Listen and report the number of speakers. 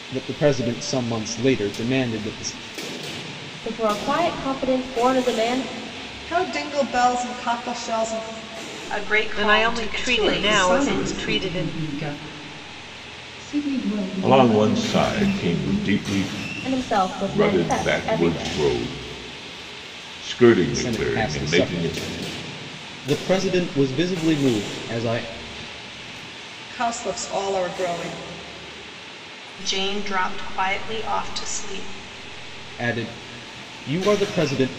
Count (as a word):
eight